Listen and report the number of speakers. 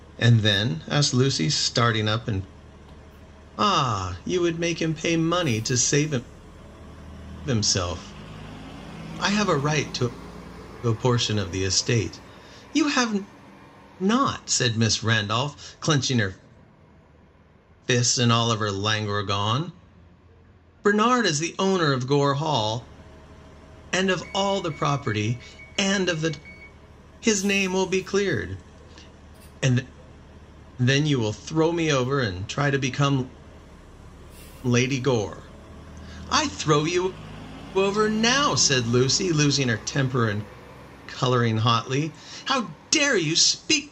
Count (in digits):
1